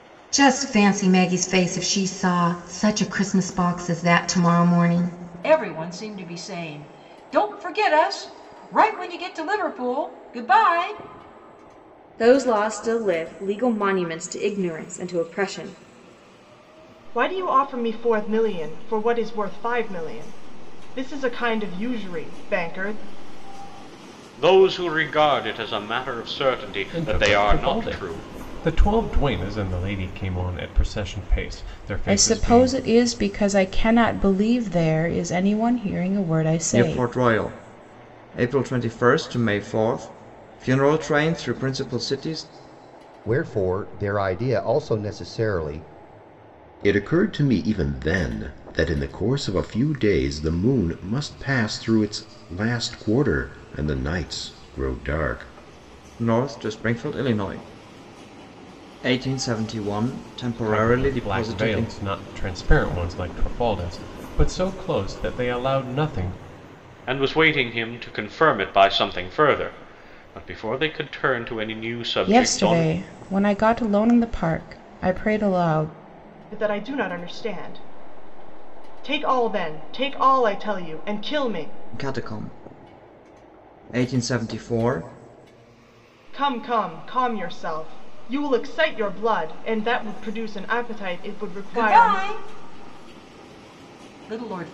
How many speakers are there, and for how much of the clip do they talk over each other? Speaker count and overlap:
10, about 5%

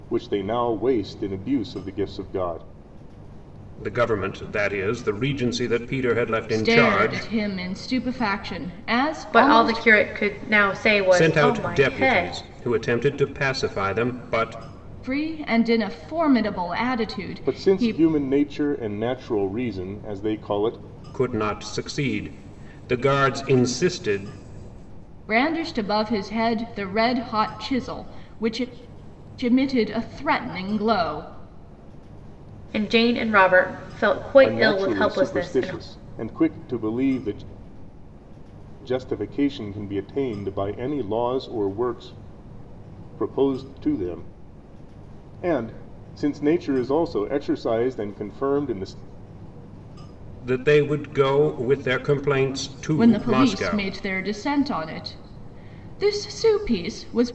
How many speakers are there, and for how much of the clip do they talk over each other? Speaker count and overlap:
4, about 10%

